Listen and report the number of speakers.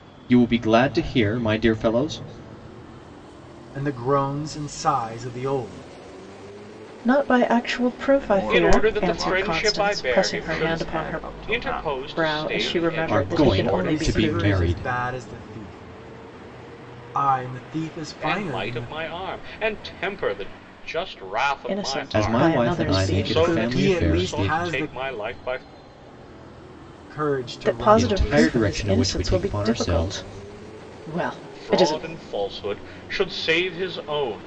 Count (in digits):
5